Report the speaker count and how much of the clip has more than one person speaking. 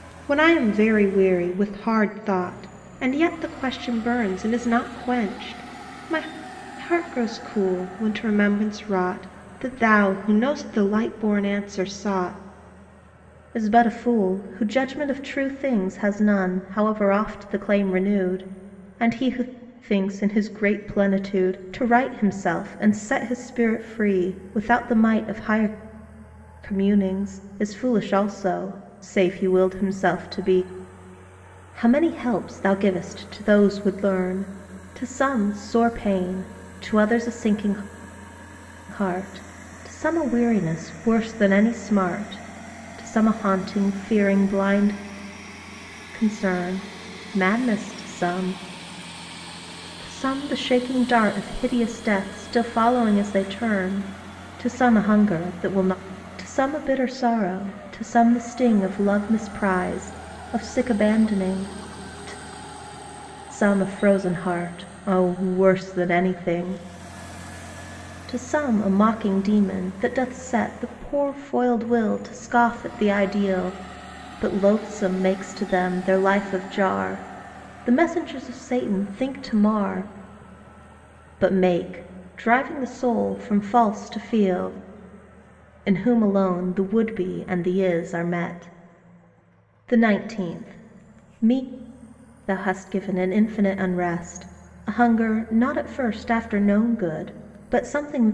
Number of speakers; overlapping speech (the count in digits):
1, no overlap